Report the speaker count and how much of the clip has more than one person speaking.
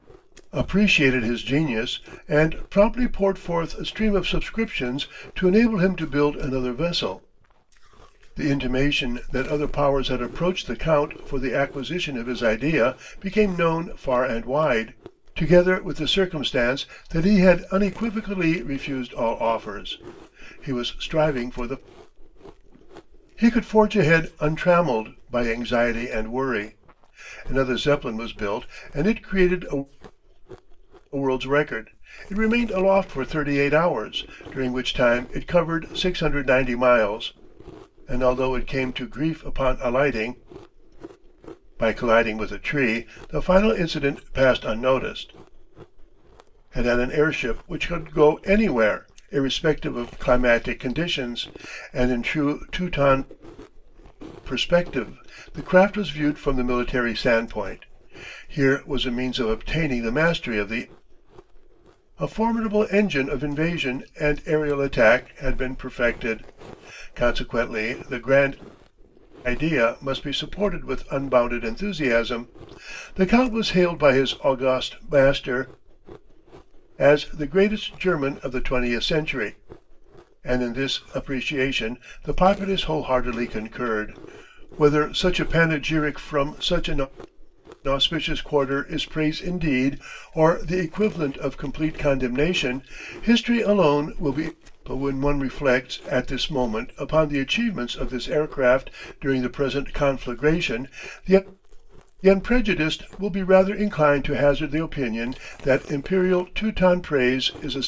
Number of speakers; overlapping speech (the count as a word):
one, no overlap